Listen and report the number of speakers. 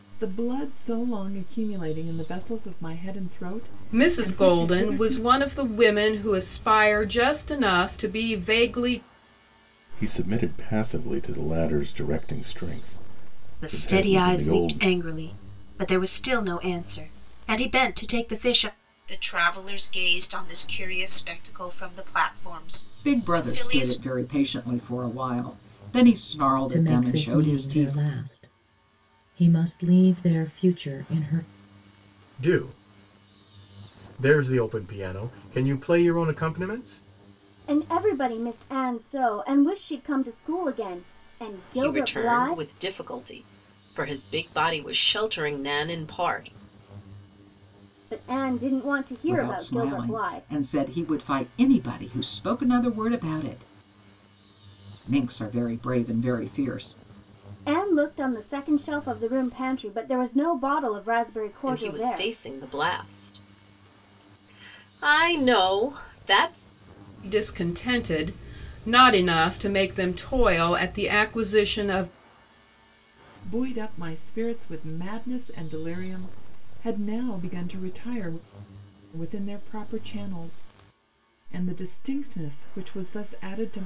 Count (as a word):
ten